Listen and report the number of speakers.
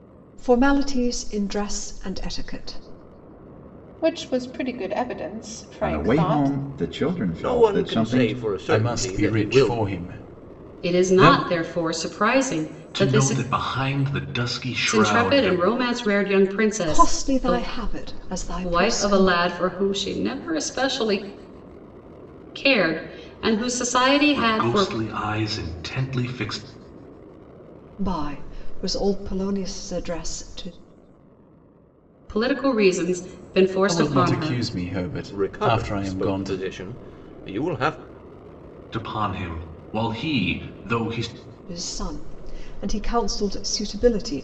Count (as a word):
seven